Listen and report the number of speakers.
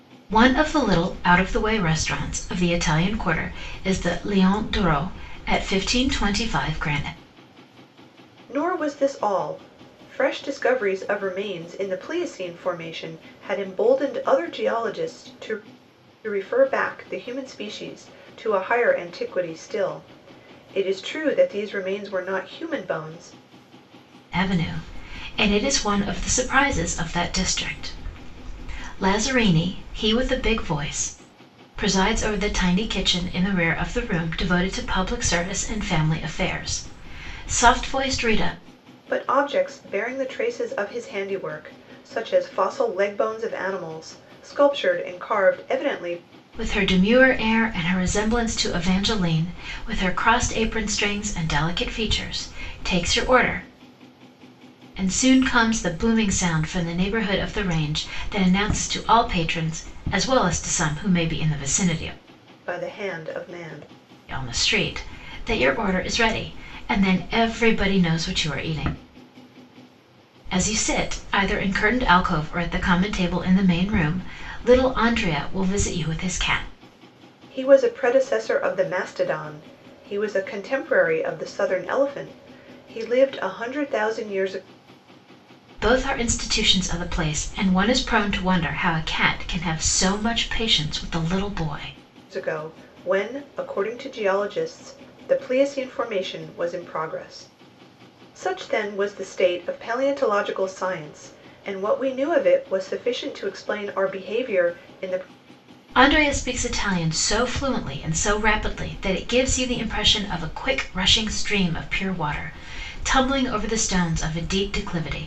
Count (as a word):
two